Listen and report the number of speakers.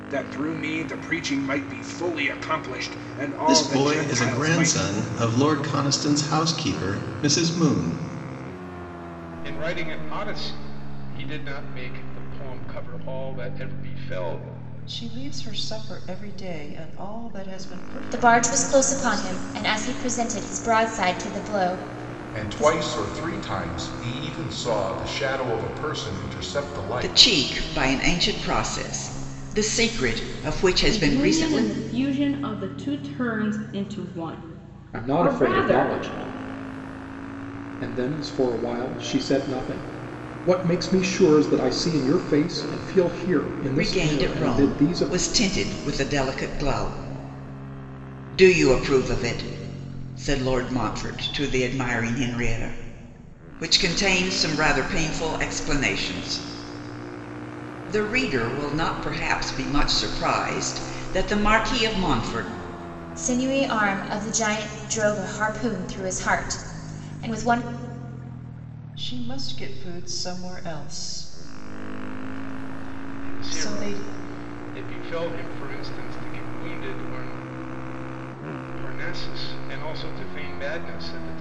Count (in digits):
9